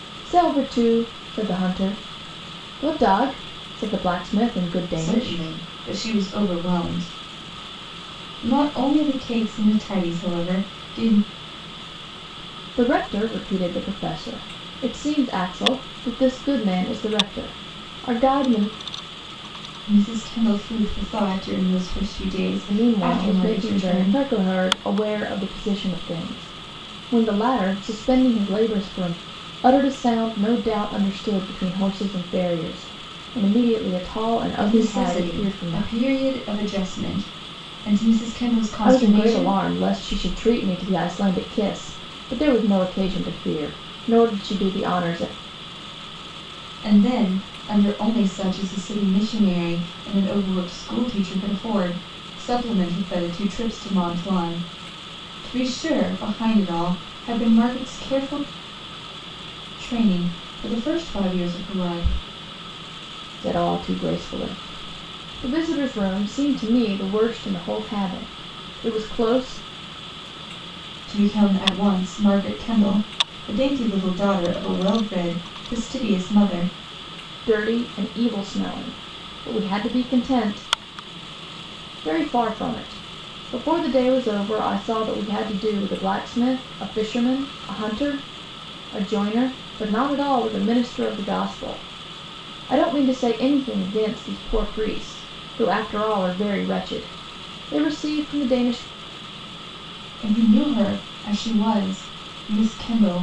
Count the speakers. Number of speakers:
two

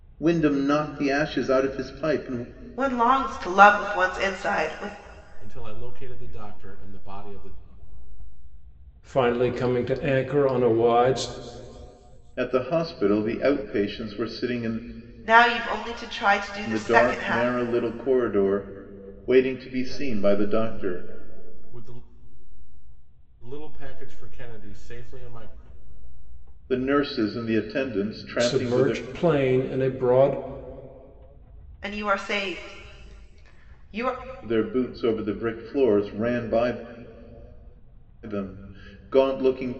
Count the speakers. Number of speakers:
four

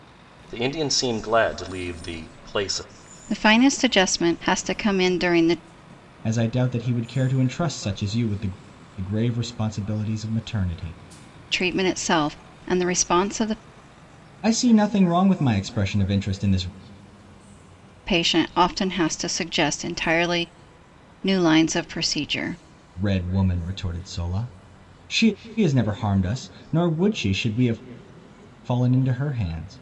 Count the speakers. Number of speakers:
three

